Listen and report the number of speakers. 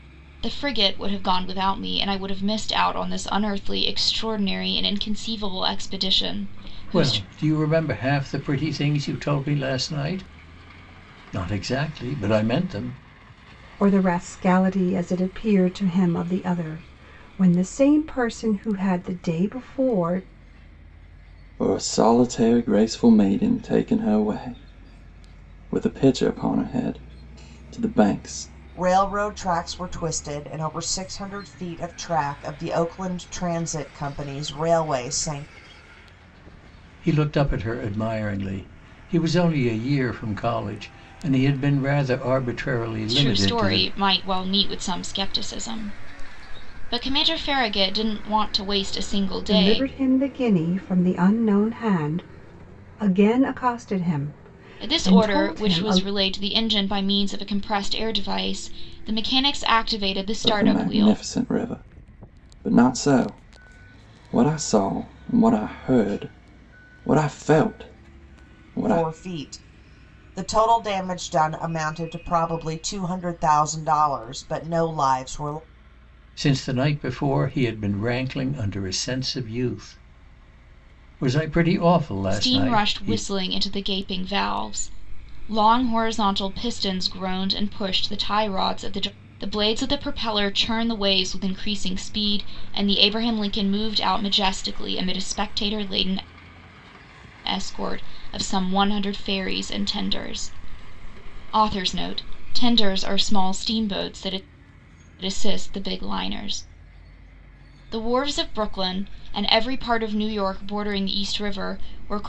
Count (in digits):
5